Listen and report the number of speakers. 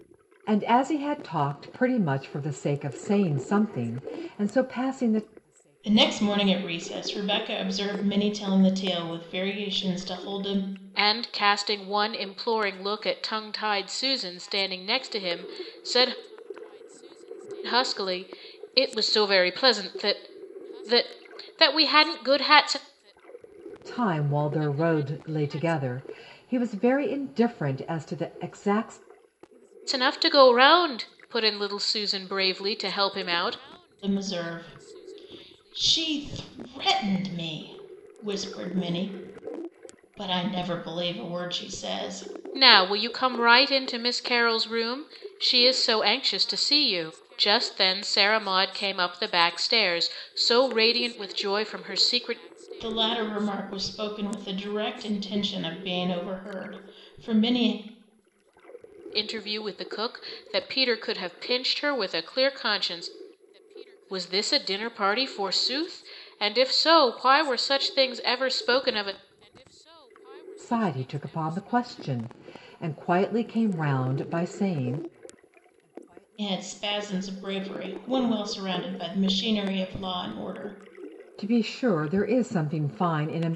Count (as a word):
three